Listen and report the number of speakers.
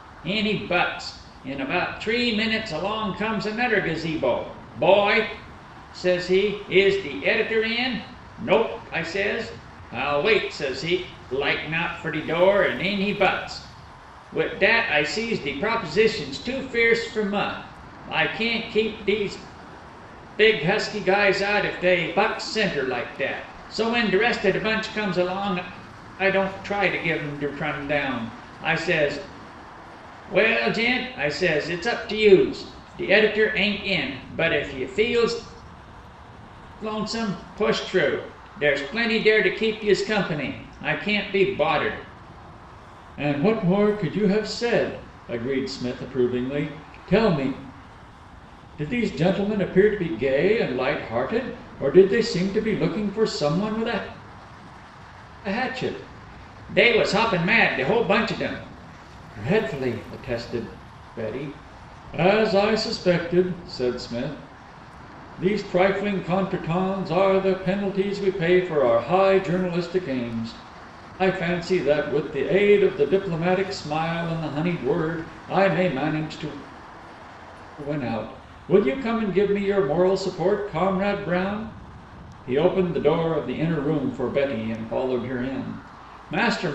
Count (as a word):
one